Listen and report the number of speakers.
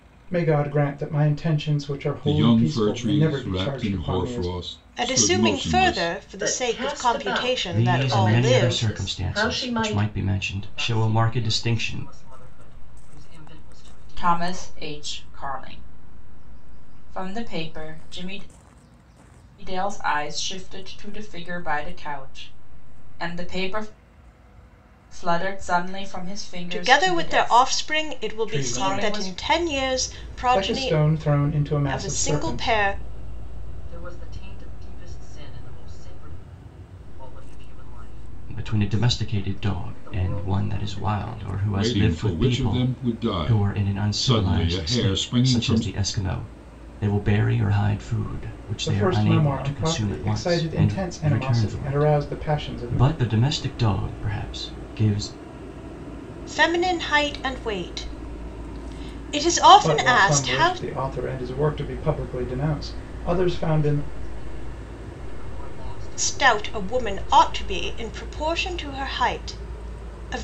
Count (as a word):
seven